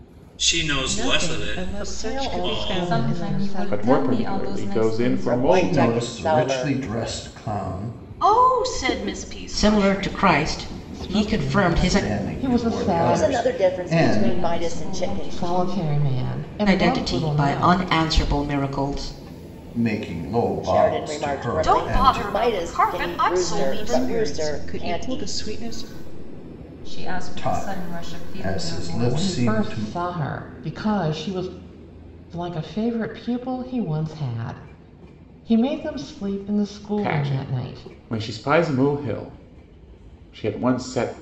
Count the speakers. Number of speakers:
9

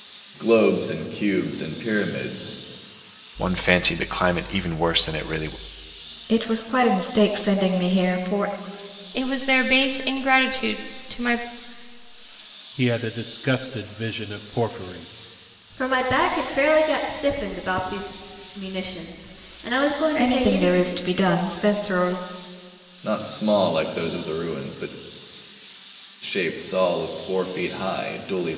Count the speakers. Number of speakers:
6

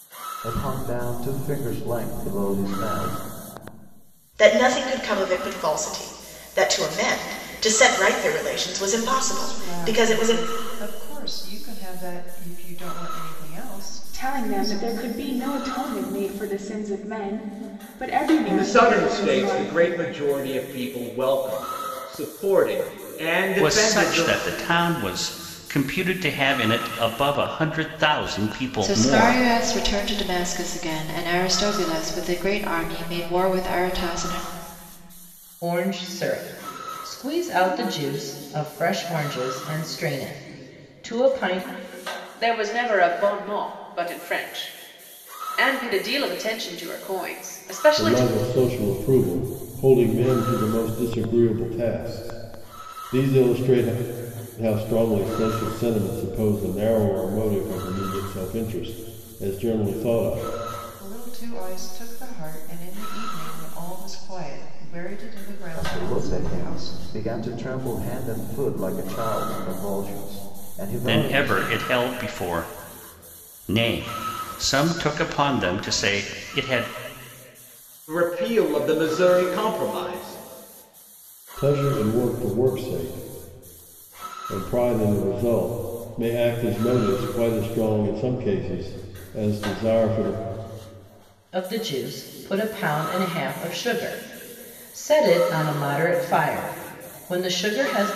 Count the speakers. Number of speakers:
10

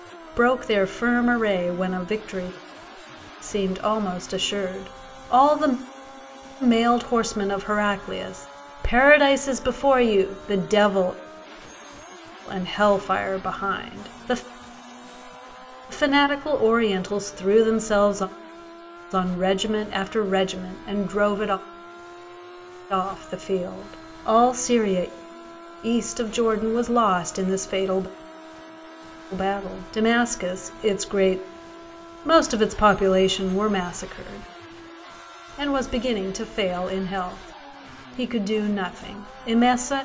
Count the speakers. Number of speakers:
1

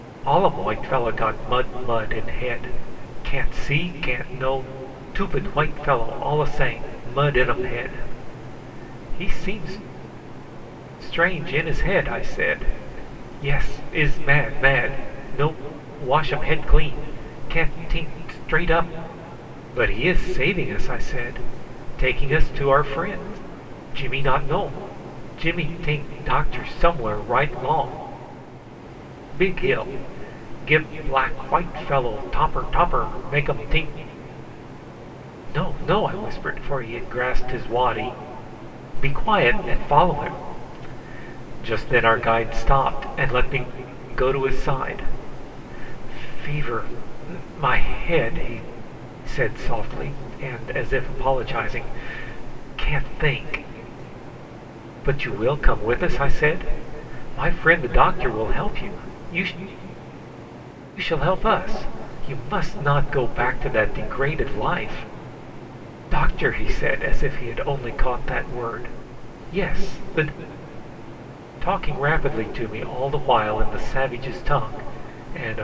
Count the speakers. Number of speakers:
1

